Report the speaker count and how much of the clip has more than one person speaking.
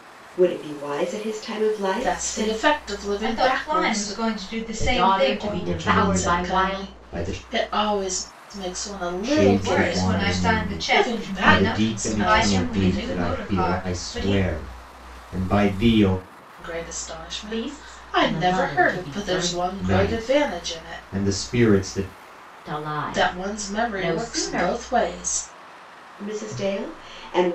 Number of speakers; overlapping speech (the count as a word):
five, about 53%